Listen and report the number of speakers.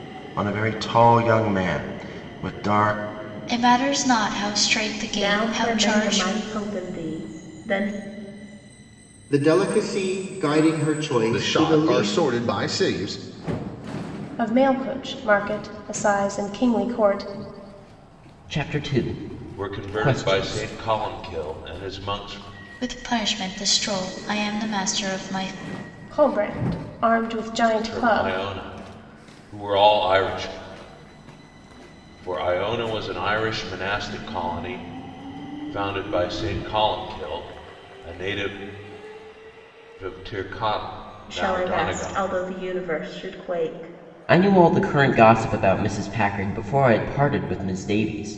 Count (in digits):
8